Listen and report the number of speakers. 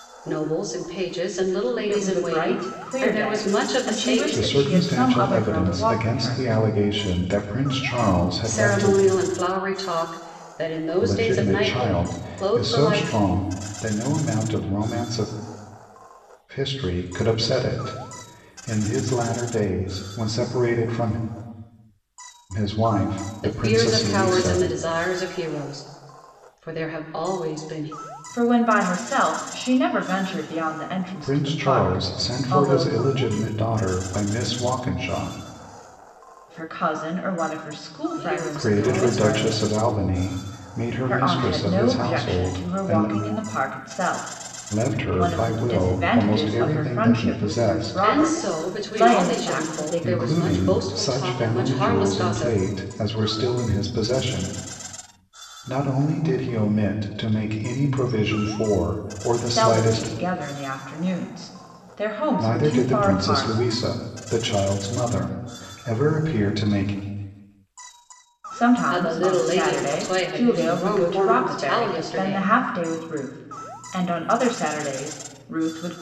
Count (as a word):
three